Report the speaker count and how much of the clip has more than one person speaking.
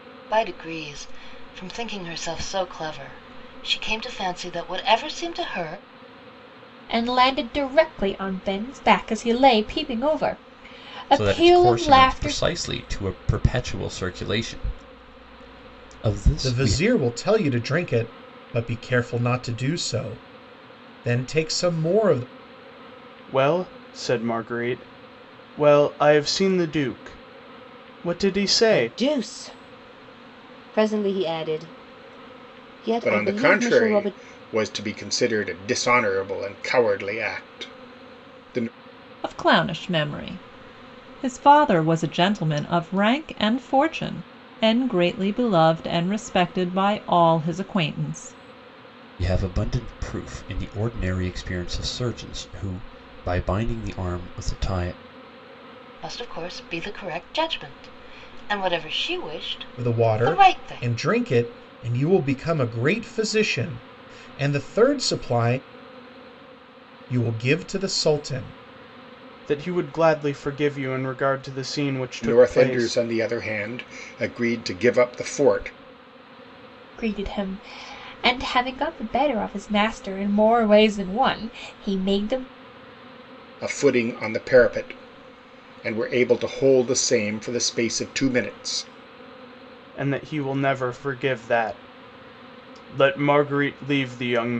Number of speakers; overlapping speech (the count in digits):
8, about 6%